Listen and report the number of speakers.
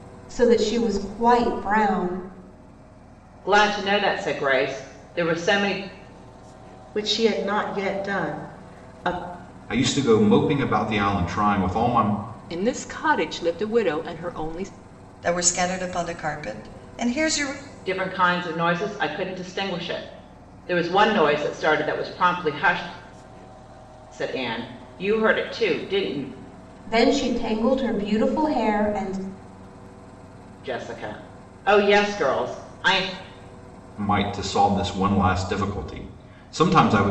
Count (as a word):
six